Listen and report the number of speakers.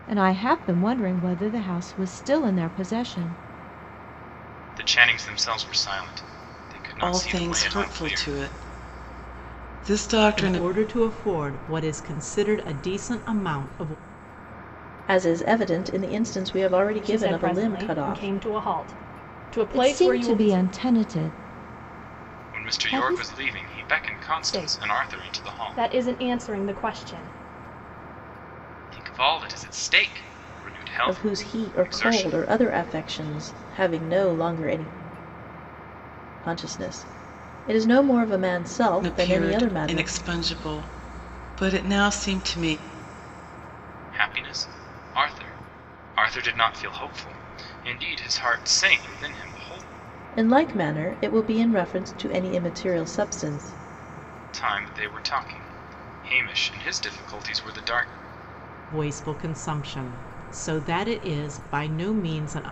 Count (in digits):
6